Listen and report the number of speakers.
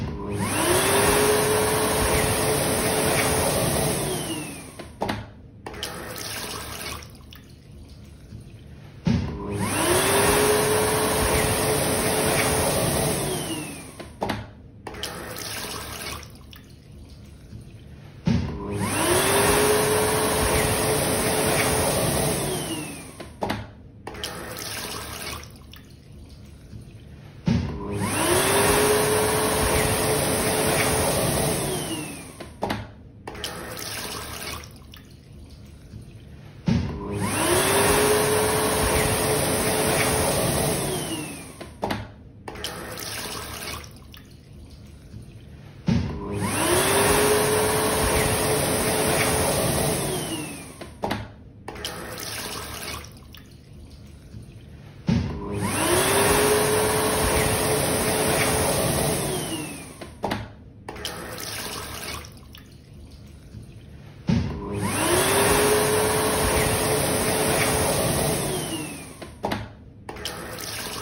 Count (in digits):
0